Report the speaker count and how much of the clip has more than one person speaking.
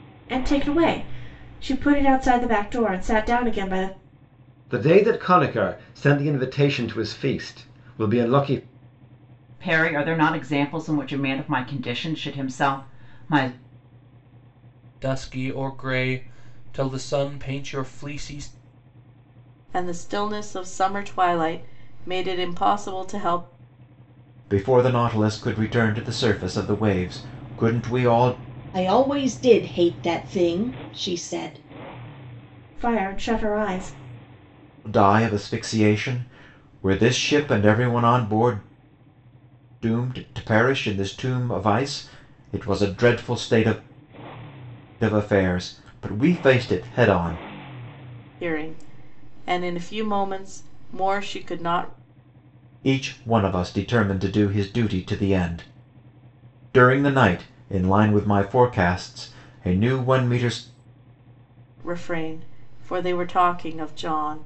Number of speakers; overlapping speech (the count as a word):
seven, no overlap